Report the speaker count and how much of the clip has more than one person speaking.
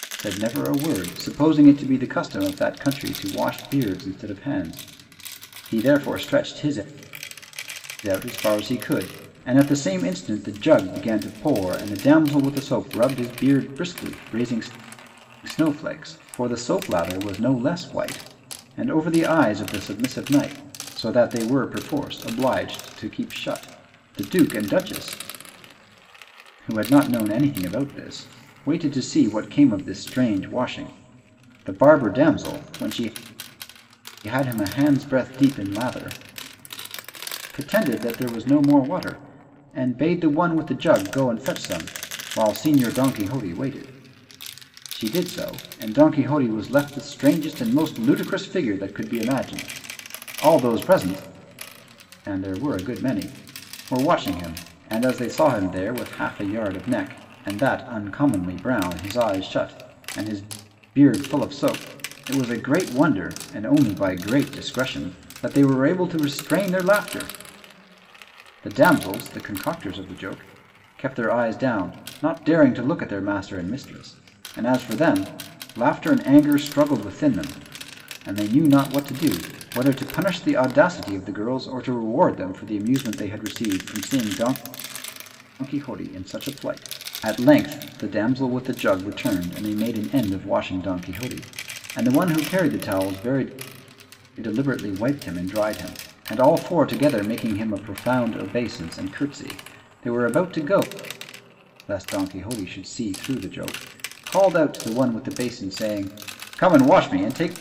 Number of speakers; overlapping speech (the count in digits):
1, no overlap